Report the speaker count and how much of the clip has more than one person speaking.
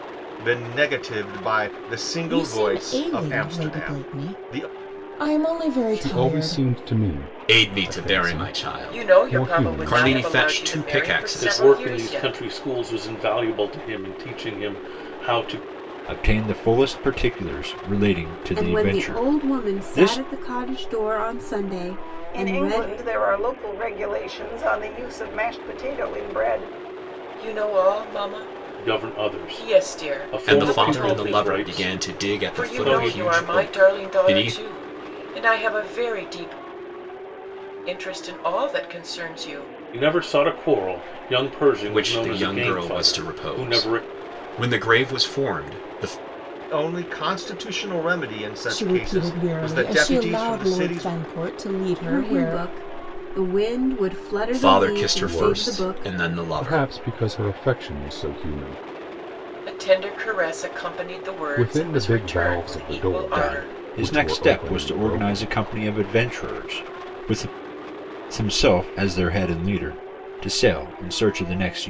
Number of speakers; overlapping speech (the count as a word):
nine, about 39%